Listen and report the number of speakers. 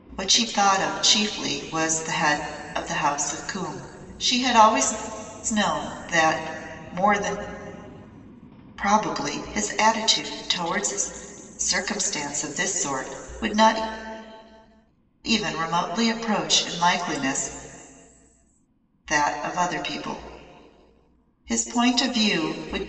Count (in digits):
1